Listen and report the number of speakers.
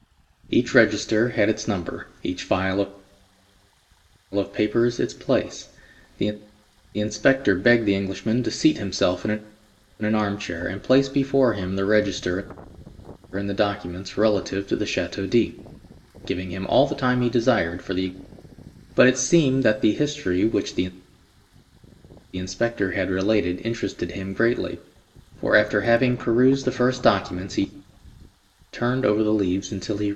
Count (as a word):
one